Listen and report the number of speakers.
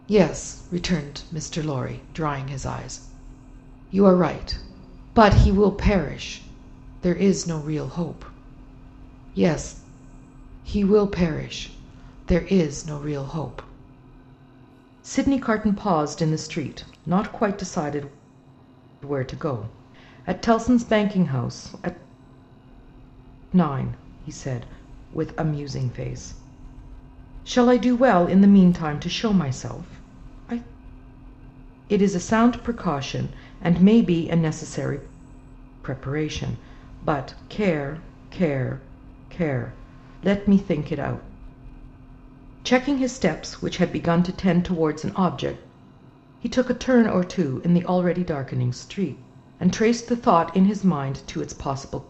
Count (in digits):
1